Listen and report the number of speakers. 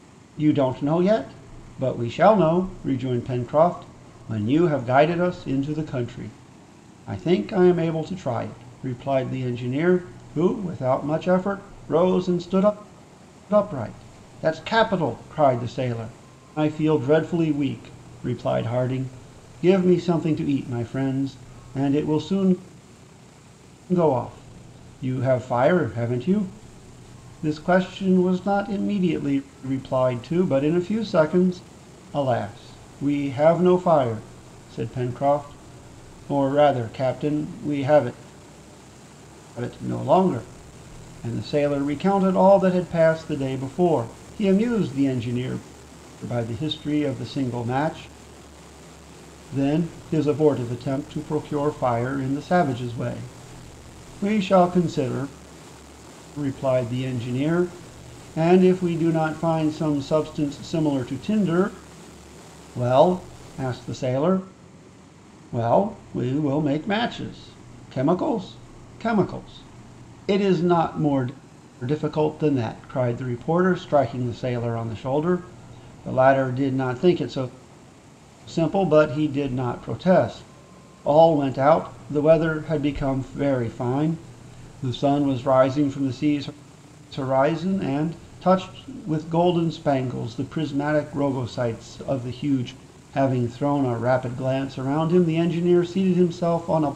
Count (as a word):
one